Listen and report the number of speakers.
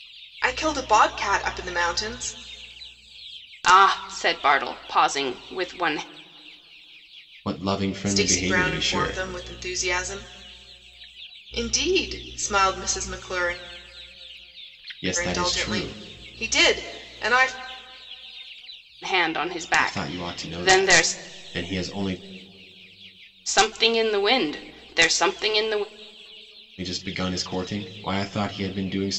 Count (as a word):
three